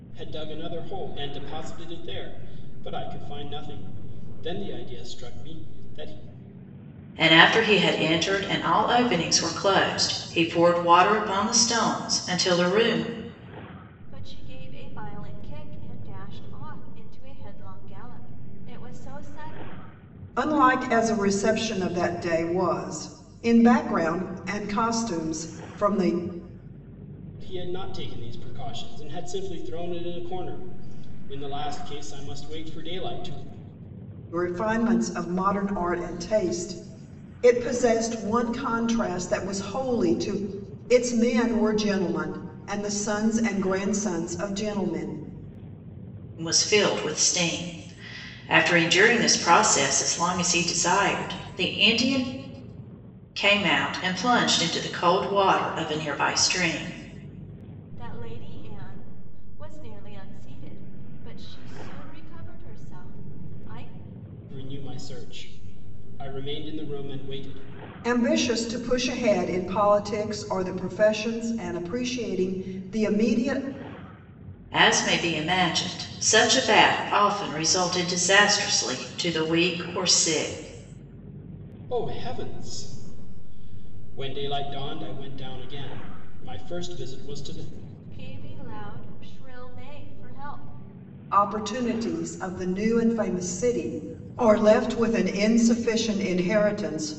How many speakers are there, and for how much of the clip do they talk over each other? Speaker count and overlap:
4, no overlap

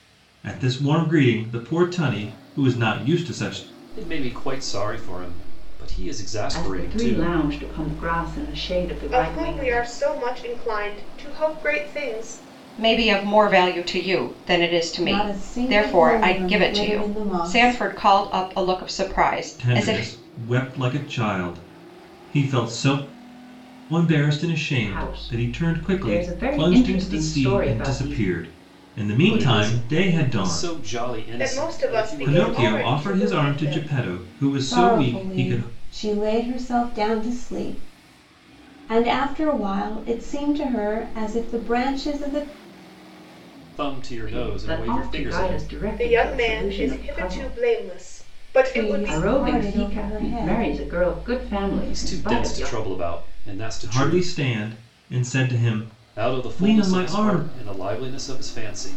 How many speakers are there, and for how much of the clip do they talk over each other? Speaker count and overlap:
6, about 37%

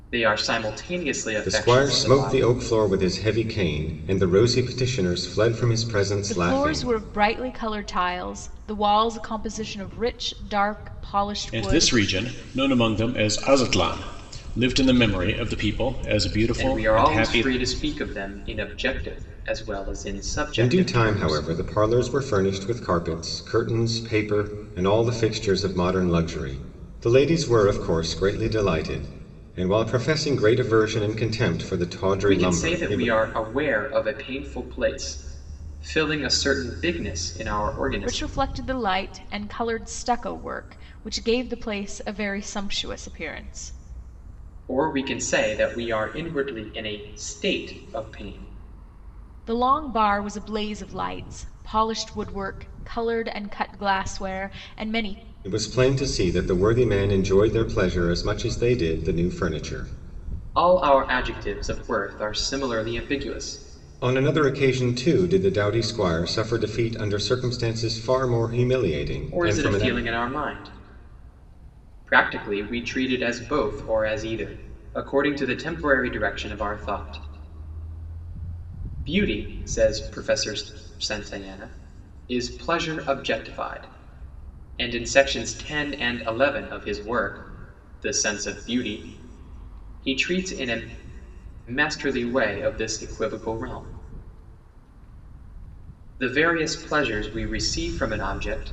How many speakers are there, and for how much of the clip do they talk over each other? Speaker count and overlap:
4, about 6%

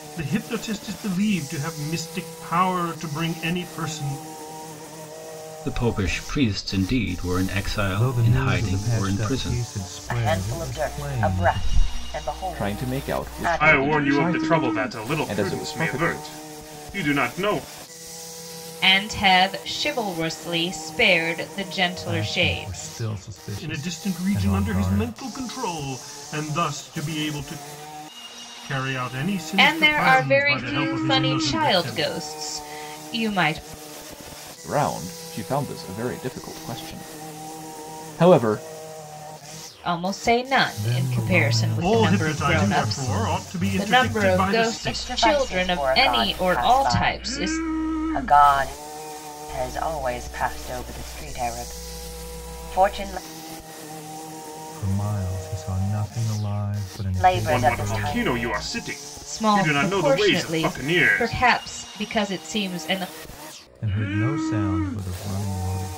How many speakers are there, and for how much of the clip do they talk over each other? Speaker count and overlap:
7, about 34%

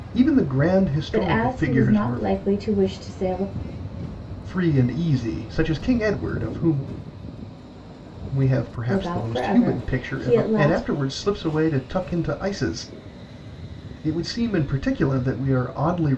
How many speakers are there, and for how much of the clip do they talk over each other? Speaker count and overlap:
2, about 20%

